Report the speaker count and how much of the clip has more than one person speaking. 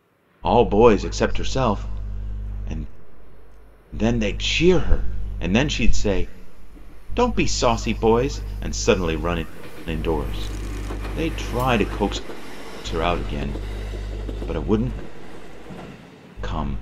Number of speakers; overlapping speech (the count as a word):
one, no overlap